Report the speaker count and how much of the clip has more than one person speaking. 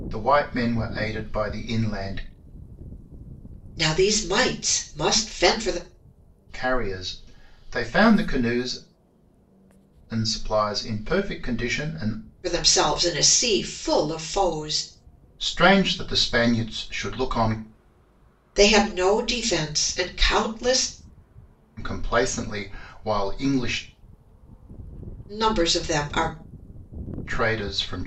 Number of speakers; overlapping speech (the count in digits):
2, no overlap